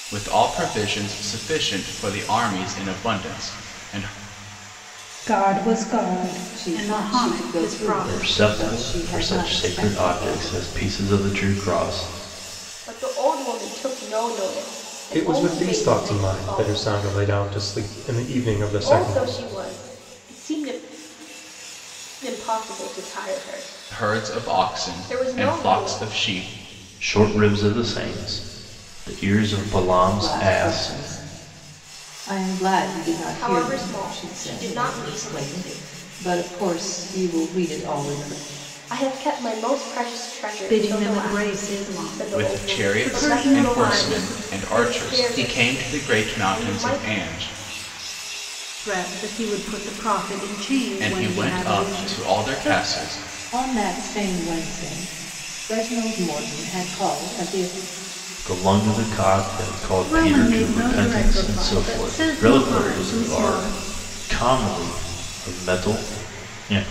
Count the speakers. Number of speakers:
six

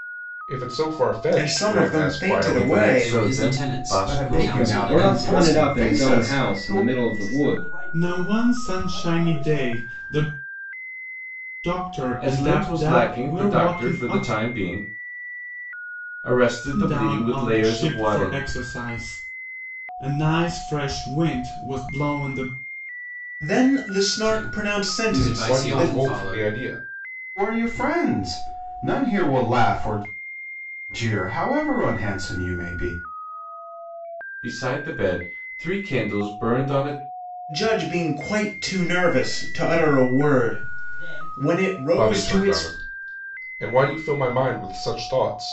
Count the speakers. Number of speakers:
eight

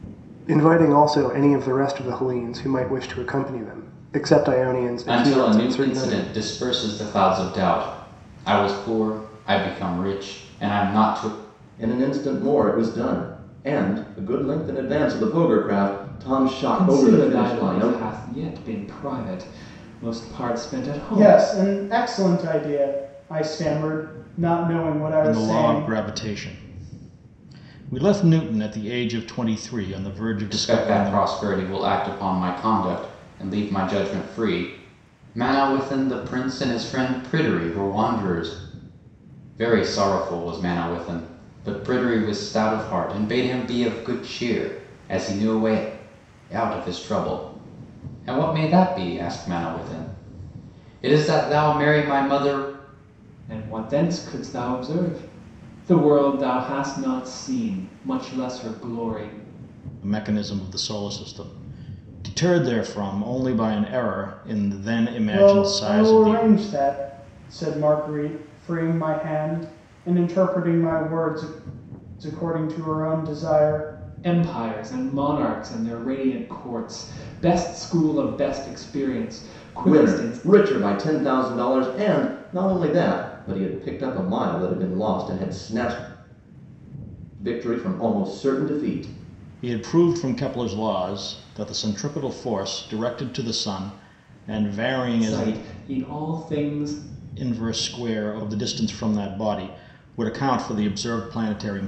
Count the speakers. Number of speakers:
six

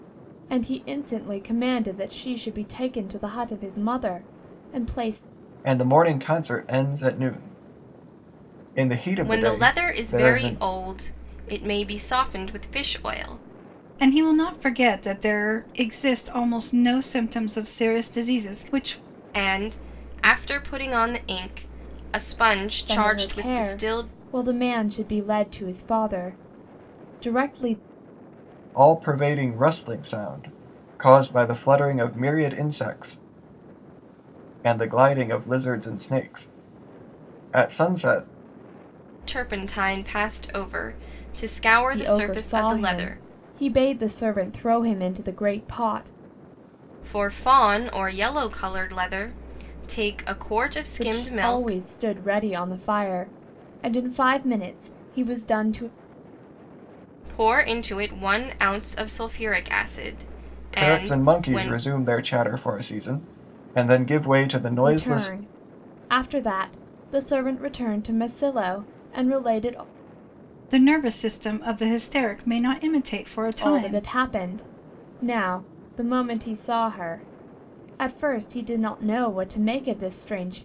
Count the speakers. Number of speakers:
four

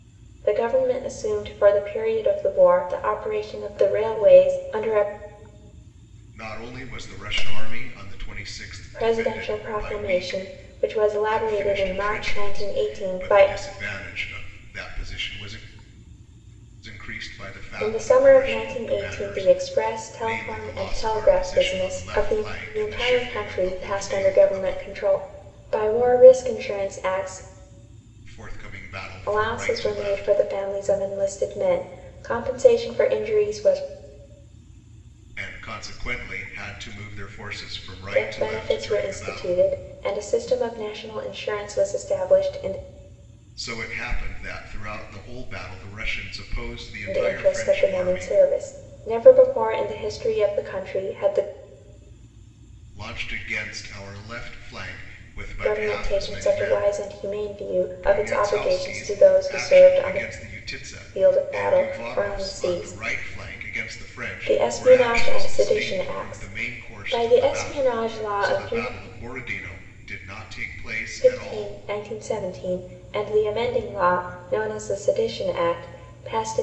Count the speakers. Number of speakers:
two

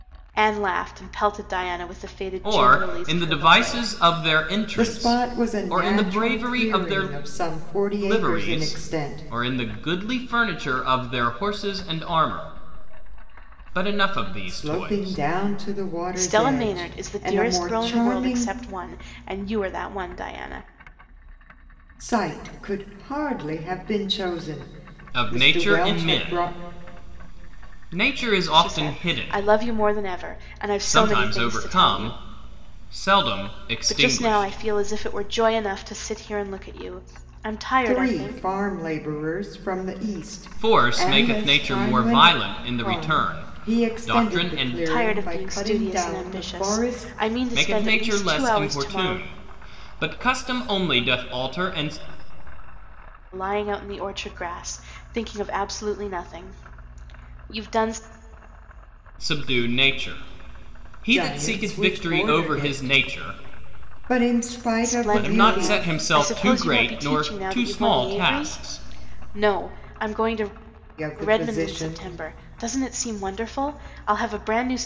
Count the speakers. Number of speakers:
three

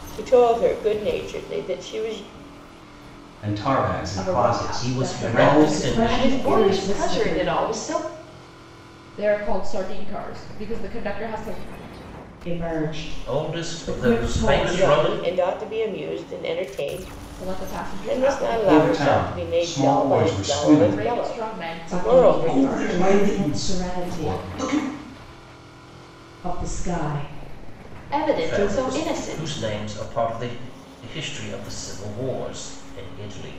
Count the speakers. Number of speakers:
six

